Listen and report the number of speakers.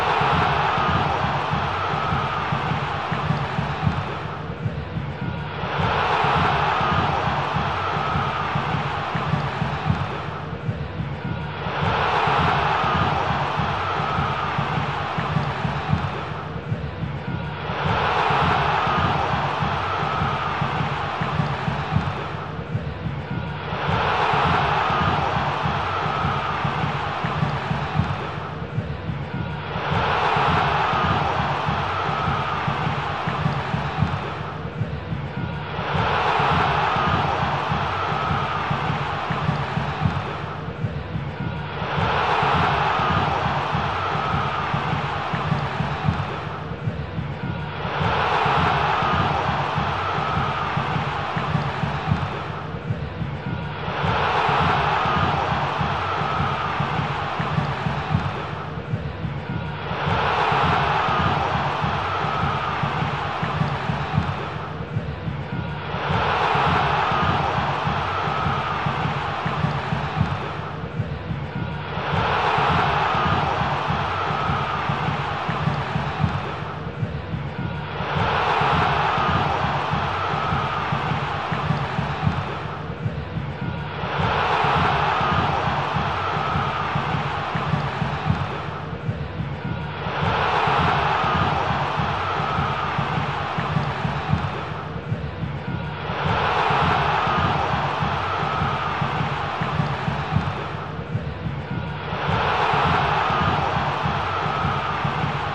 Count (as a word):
zero